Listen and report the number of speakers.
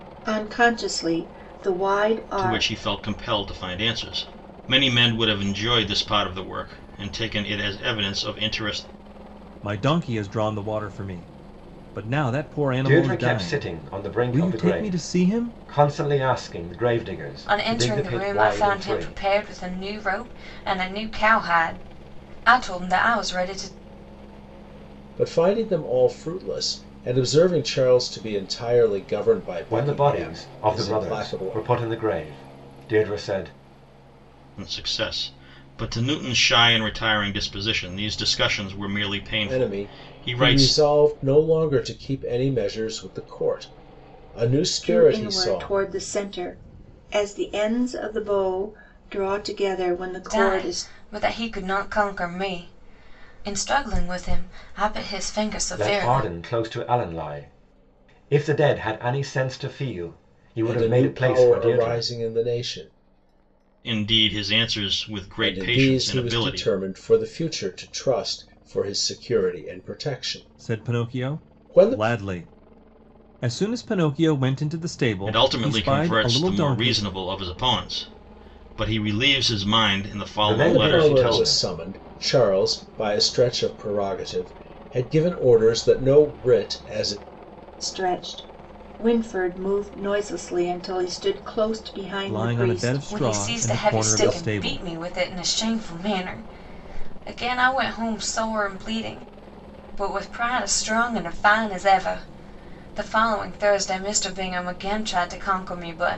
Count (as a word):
six